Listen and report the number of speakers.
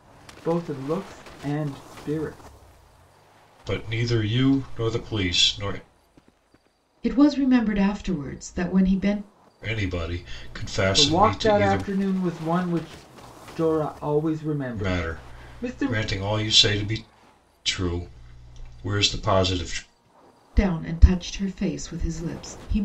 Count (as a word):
three